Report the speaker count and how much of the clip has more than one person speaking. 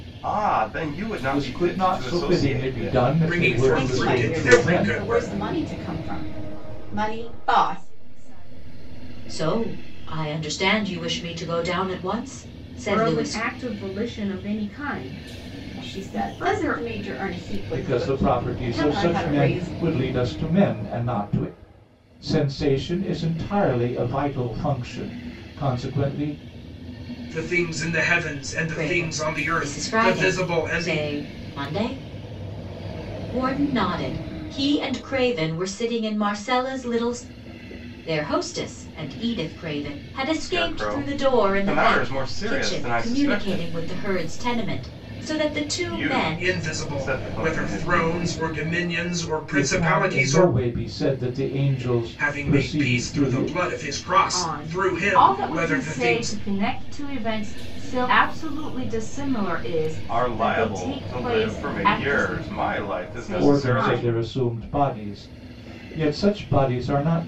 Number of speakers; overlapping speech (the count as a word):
seven, about 46%